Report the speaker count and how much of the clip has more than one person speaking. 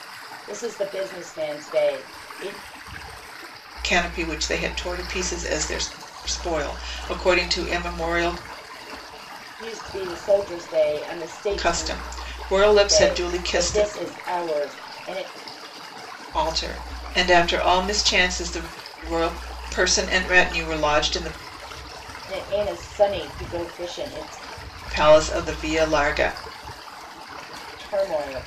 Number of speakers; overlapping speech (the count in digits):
2, about 6%